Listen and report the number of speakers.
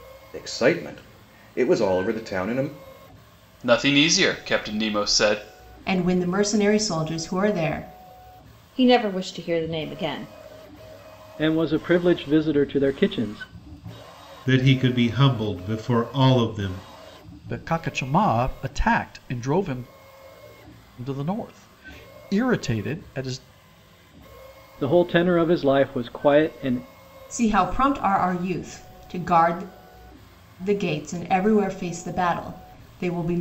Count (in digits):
7